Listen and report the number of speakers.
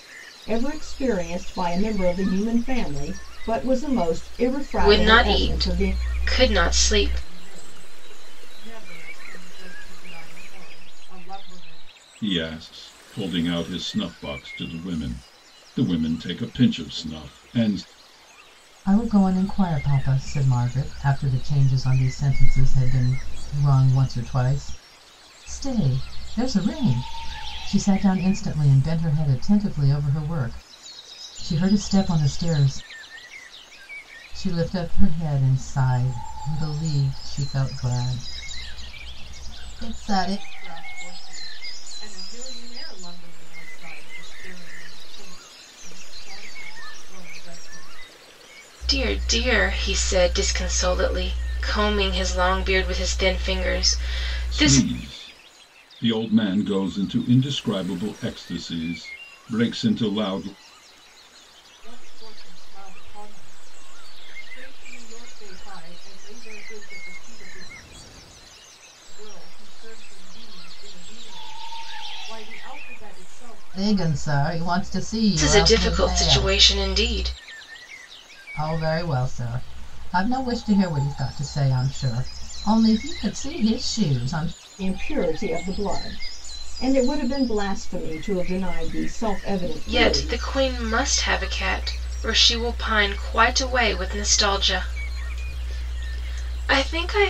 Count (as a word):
five